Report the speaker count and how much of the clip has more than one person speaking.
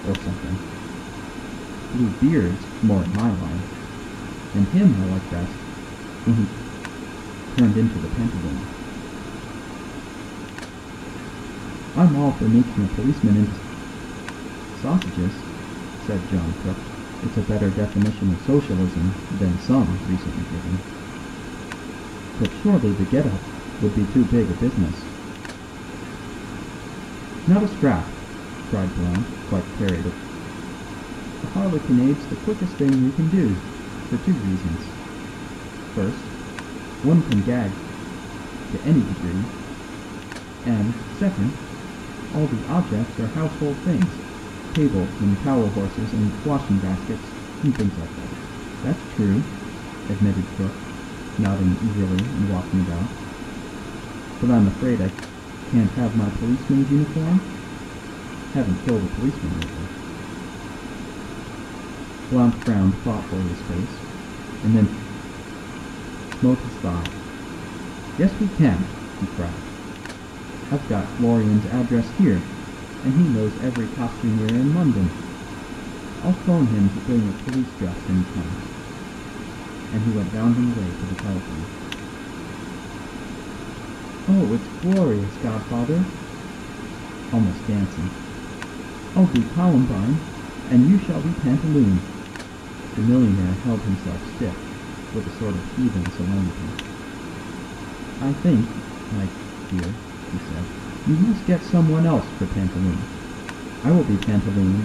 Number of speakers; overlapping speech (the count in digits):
1, no overlap